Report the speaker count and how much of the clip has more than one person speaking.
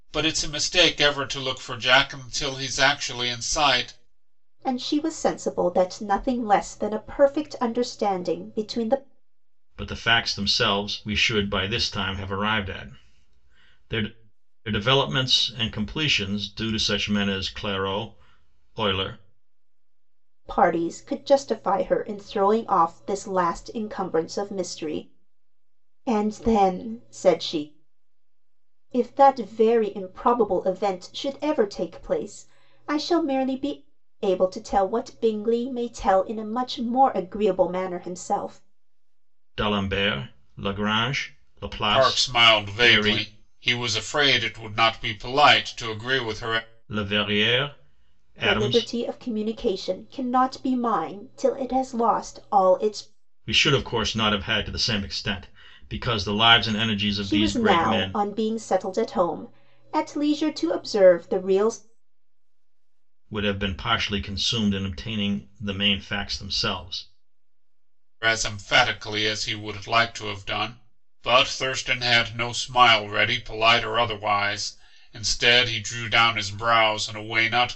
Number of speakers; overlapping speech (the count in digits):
3, about 4%